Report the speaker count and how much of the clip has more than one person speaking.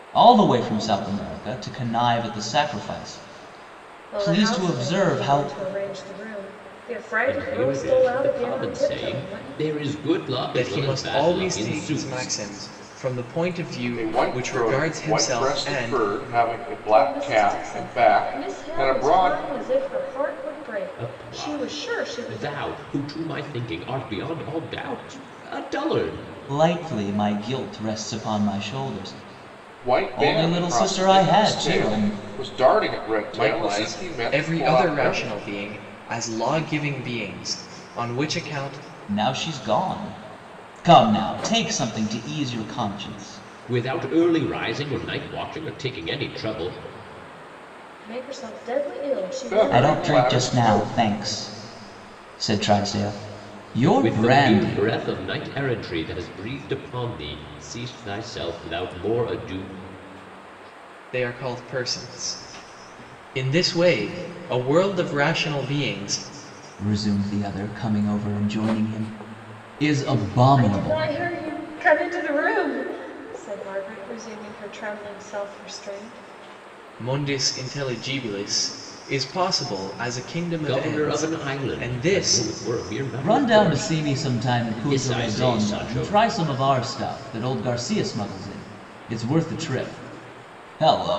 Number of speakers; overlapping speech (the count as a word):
five, about 26%